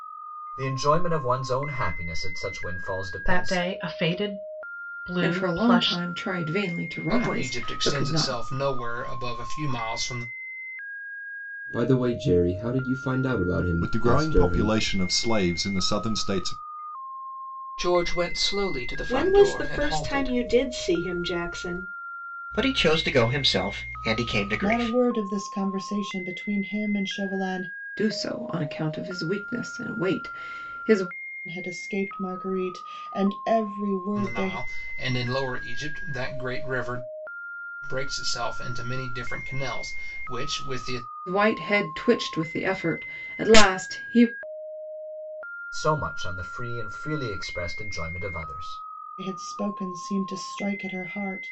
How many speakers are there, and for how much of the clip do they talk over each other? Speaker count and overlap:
10, about 11%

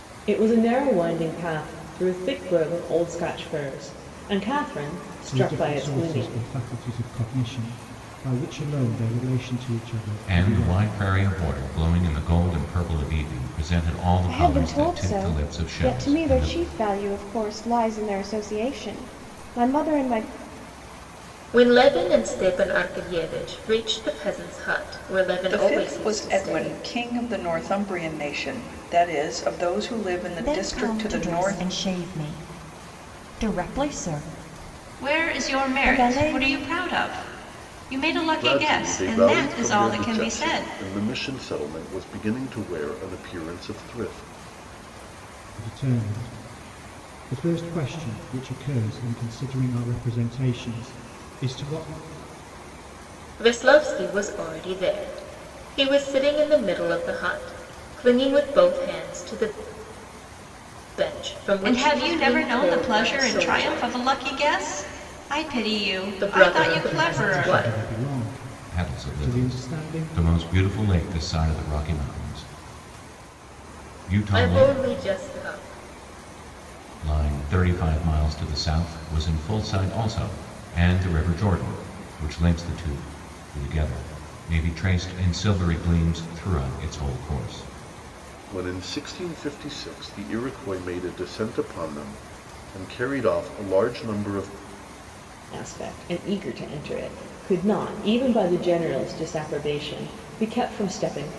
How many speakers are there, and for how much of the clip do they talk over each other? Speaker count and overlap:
9, about 17%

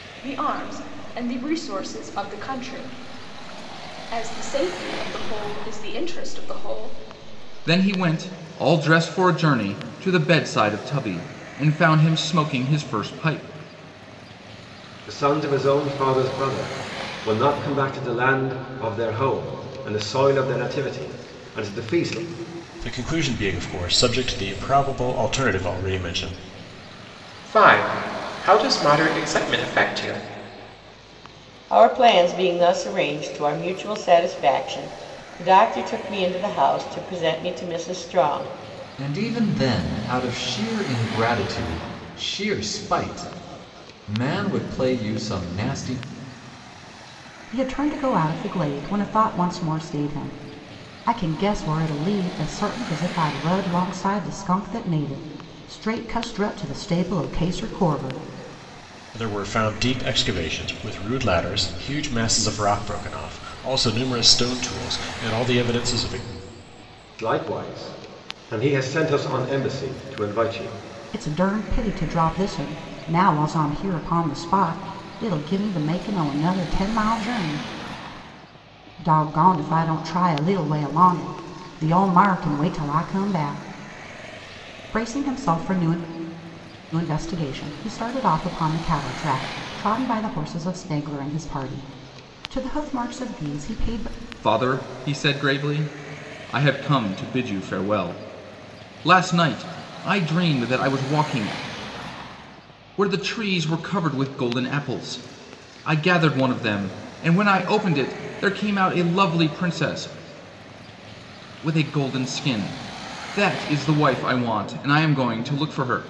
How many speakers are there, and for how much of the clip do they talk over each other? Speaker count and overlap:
8, no overlap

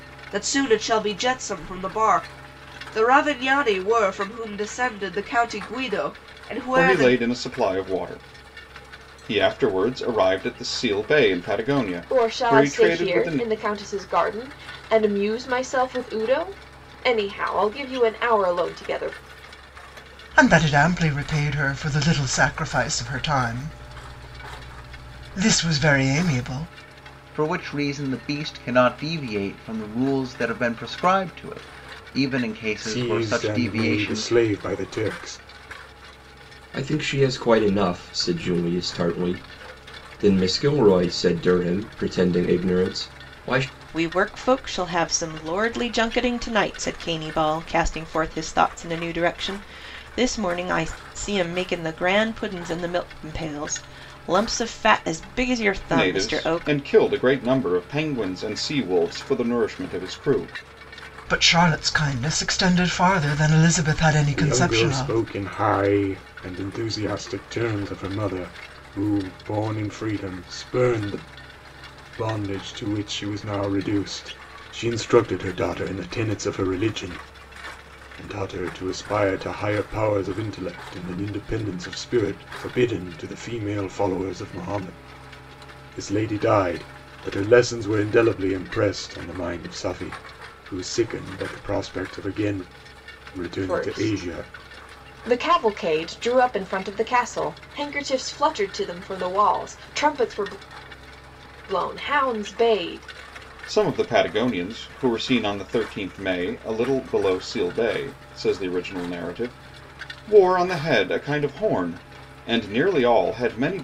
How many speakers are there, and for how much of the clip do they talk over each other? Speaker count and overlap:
8, about 5%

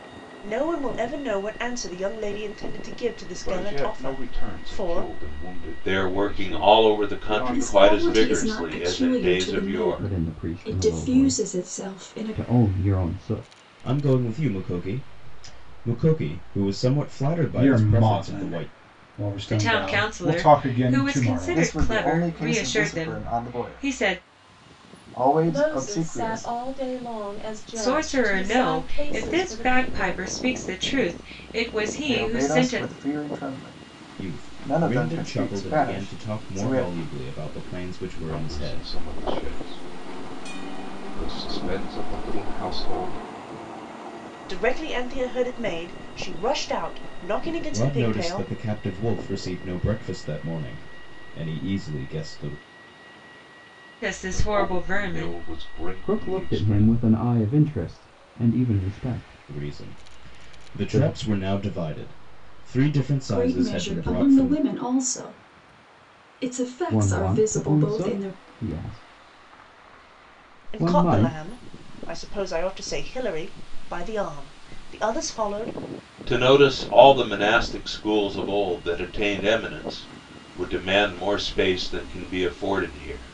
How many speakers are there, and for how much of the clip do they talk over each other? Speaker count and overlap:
10, about 37%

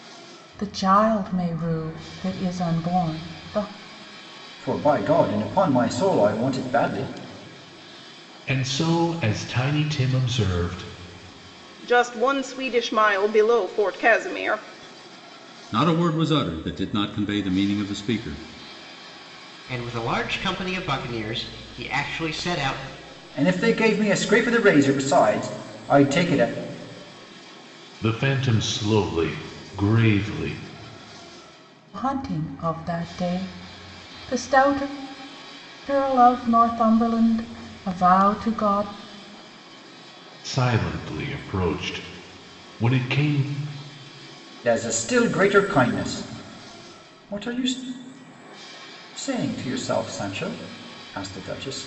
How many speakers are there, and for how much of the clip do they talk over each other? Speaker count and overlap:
6, no overlap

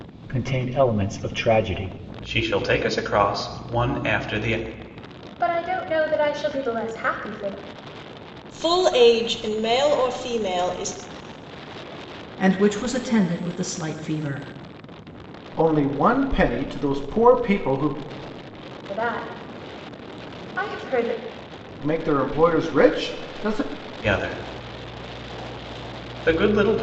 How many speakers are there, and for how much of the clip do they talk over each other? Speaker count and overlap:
6, no overlap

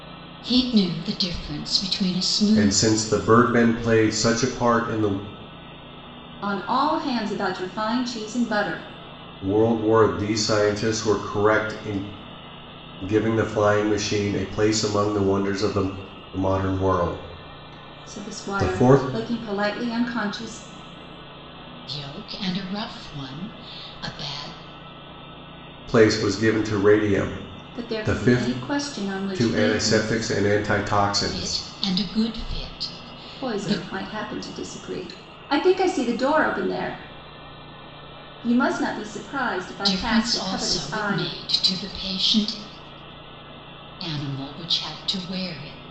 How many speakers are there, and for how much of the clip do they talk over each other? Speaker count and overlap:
3, about 13%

